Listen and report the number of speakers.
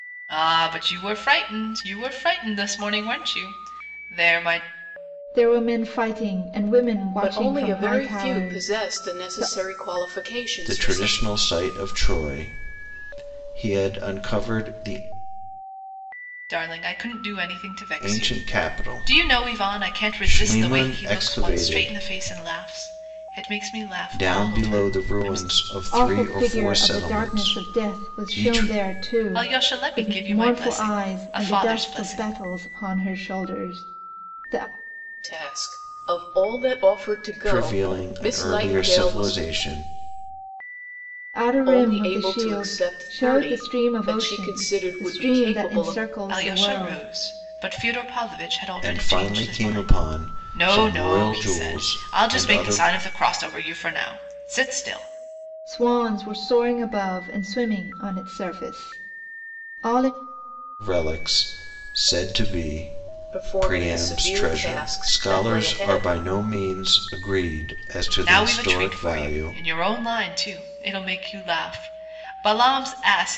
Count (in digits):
4